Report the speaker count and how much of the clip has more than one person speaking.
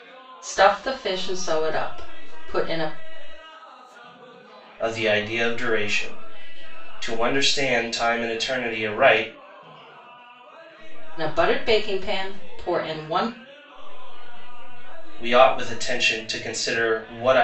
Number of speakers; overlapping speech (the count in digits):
3, about 36%